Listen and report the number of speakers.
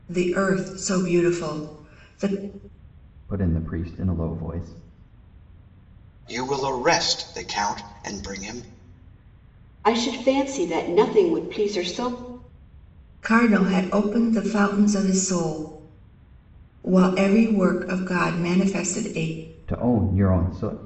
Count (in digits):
4